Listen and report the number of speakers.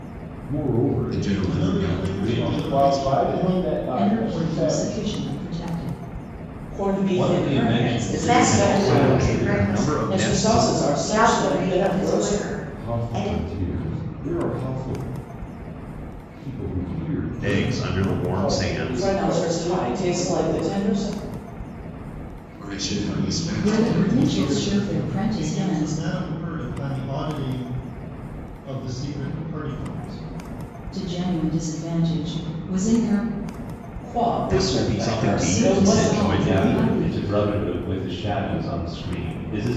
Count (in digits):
9